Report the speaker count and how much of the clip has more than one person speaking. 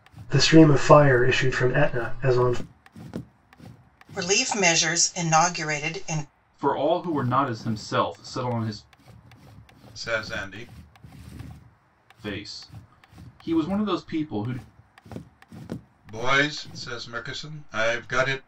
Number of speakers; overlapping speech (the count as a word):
four, no overlap